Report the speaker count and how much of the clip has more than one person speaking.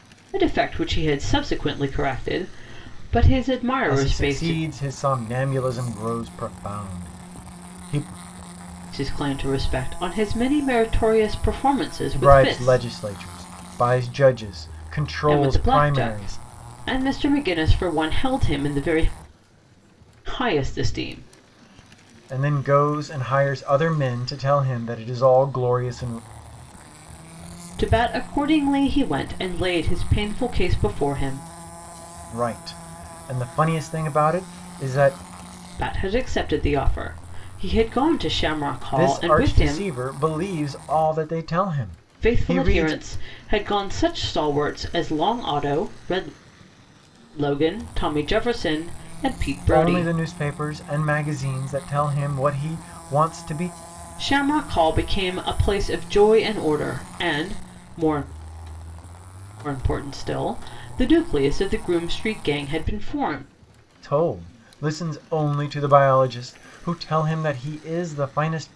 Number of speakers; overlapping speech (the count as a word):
two, about 7%